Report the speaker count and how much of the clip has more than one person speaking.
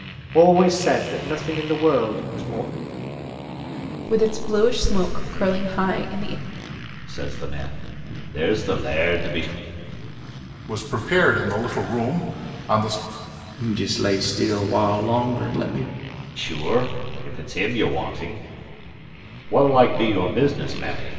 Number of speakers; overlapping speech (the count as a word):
five, no overlap